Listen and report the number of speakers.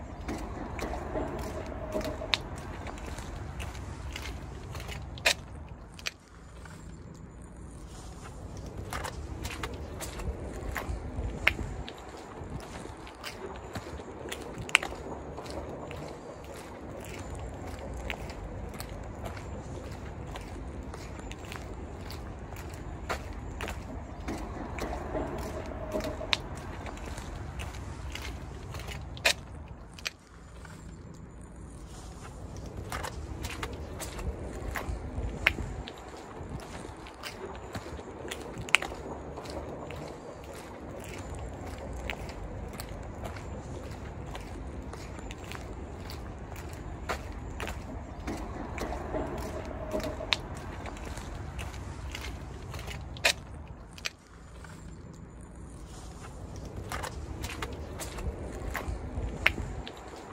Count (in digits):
0